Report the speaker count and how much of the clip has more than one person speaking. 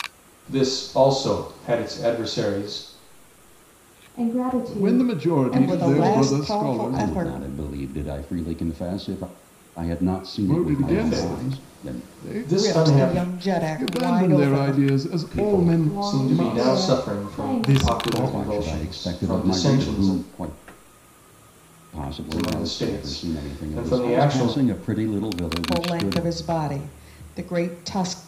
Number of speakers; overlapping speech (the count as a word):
five, about 51%